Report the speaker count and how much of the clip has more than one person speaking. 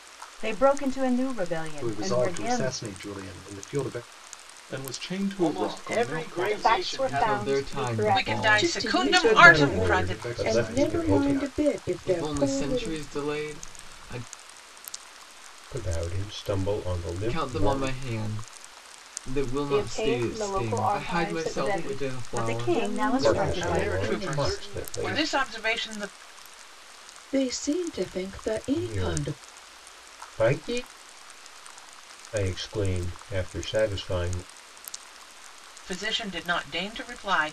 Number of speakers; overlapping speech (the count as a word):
nine, about 42%